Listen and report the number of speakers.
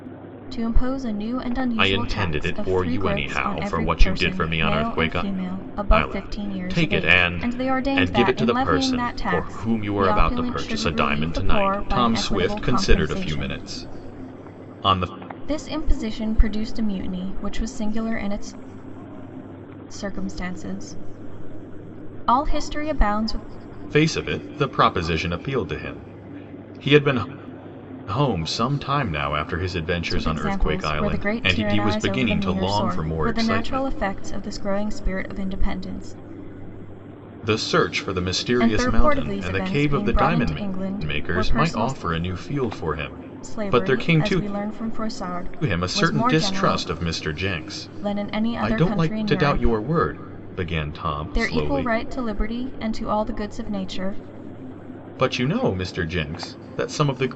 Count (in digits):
2